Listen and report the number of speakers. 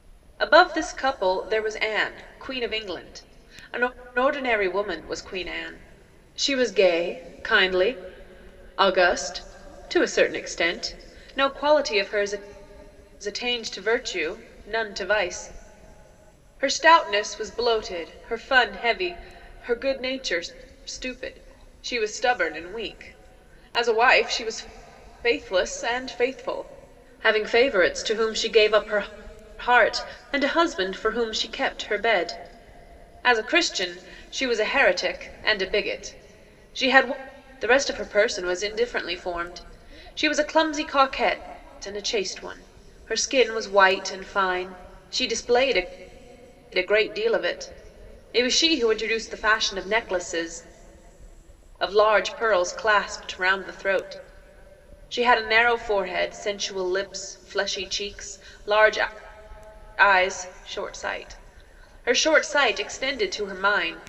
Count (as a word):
one